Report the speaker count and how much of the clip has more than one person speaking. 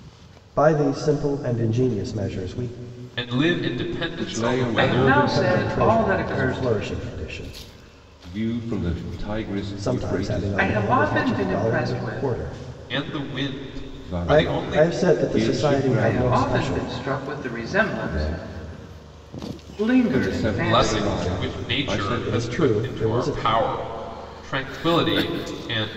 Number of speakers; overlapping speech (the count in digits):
4, about 51%